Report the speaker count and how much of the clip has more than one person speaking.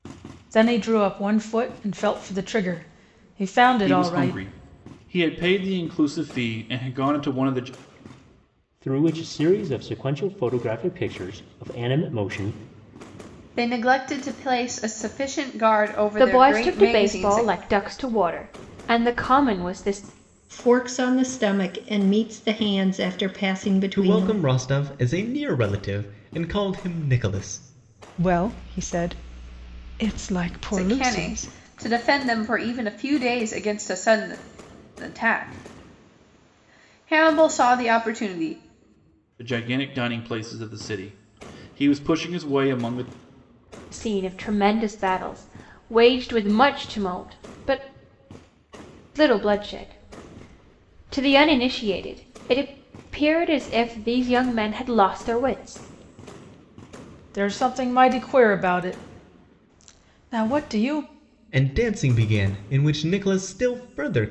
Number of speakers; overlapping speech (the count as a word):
eight, about 5%